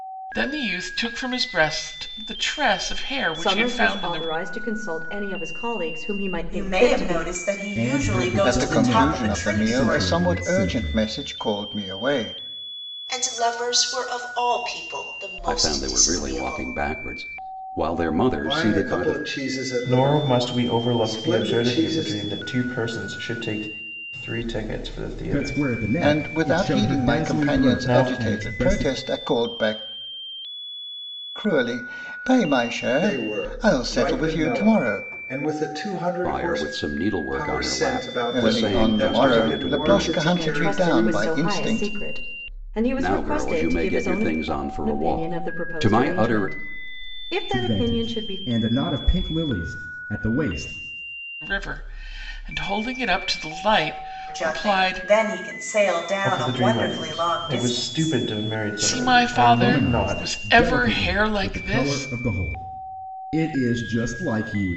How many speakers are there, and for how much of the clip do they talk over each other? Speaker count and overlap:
nine, about 47%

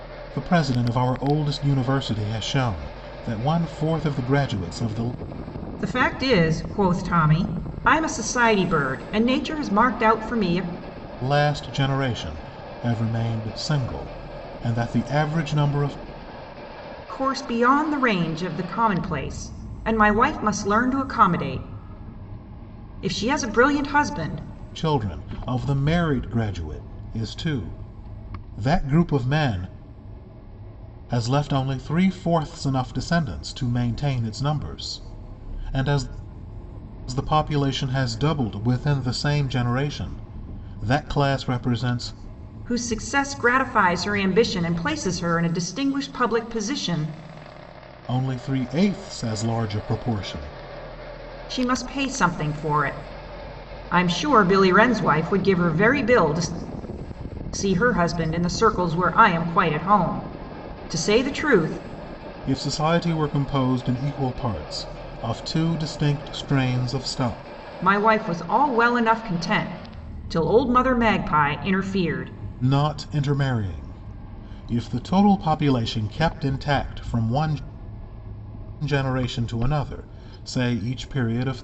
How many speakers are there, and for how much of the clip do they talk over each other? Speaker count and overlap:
two, no overlap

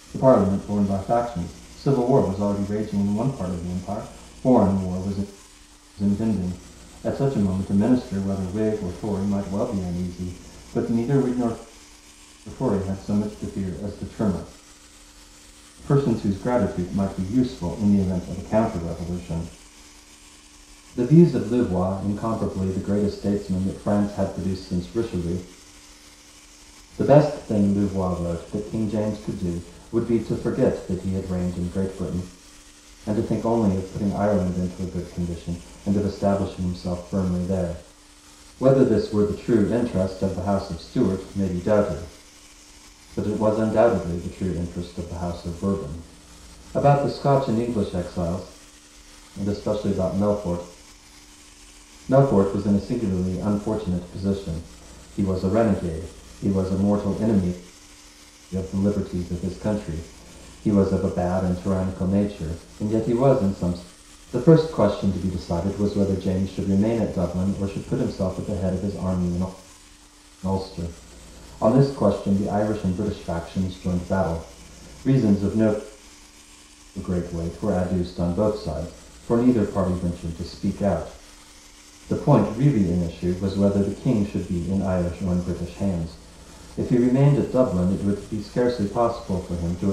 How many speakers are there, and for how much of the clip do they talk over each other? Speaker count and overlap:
one, no overlap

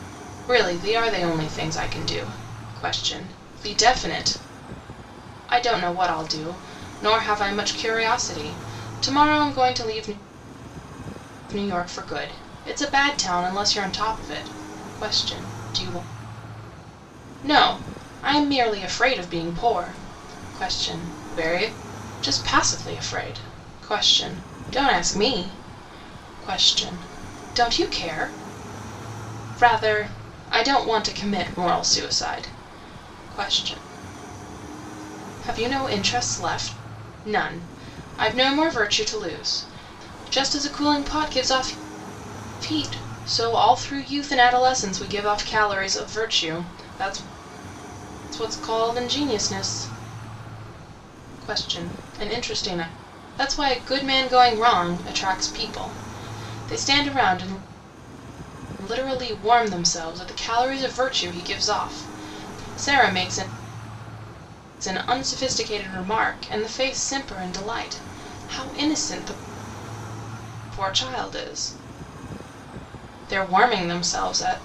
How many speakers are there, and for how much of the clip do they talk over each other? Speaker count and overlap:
one, no overlap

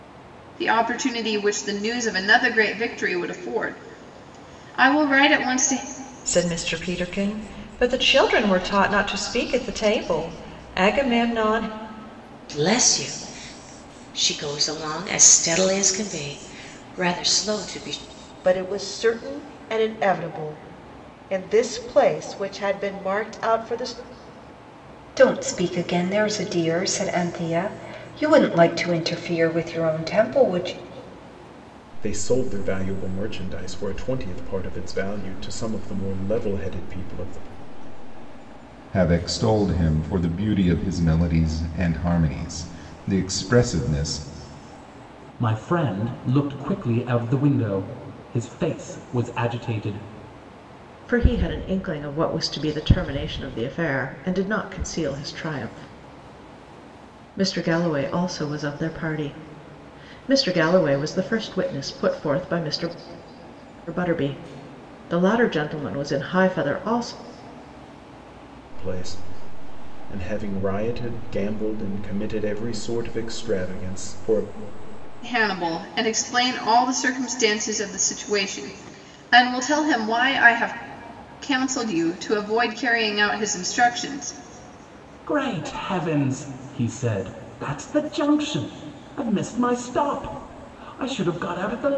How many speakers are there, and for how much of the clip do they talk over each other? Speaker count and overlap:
nine, no overlap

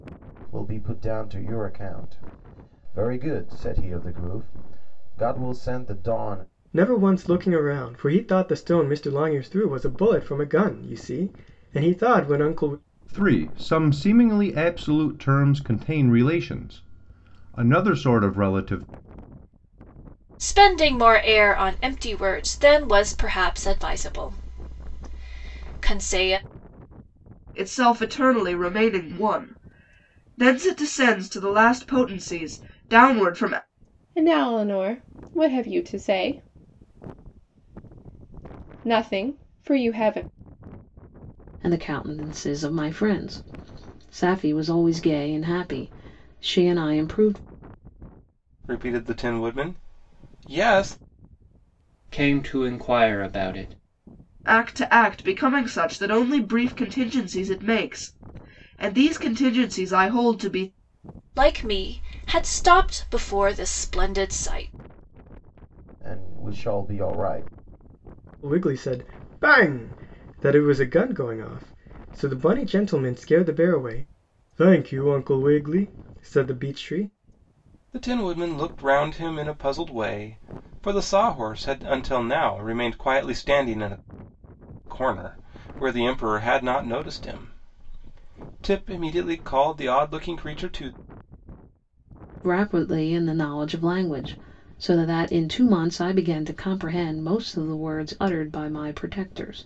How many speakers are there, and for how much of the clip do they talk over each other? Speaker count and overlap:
nine, no overlap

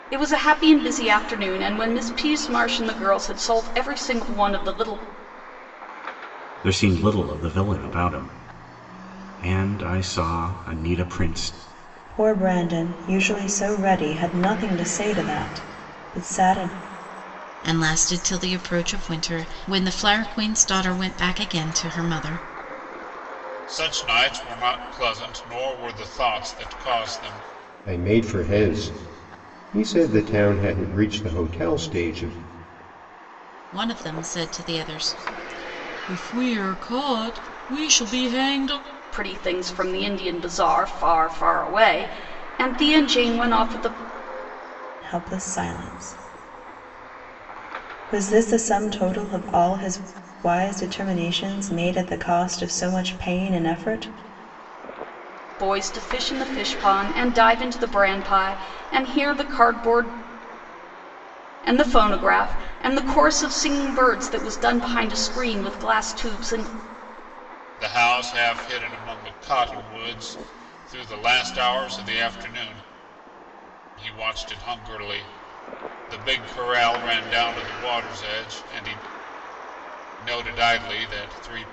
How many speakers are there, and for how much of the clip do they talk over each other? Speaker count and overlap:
six, no overlap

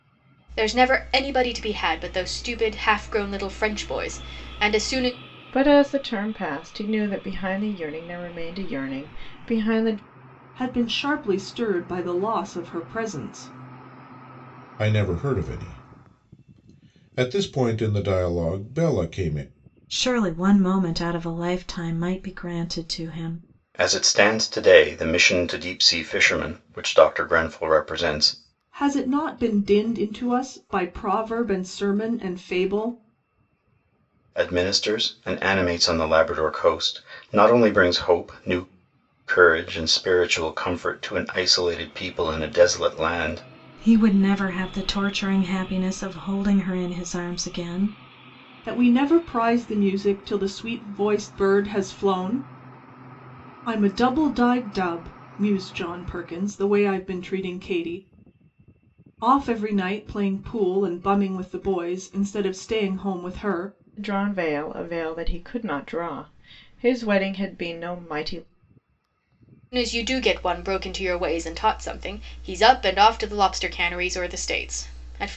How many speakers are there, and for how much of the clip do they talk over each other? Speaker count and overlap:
six, no overlap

